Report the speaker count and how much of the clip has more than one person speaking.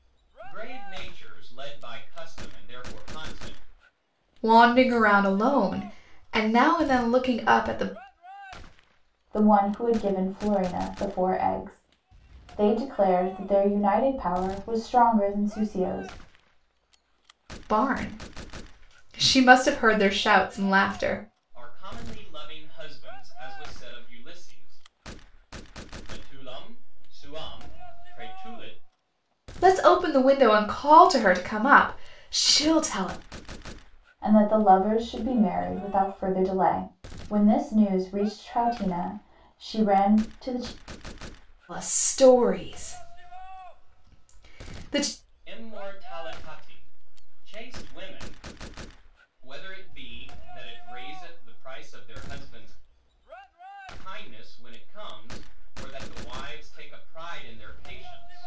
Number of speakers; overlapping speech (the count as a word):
three, no overlap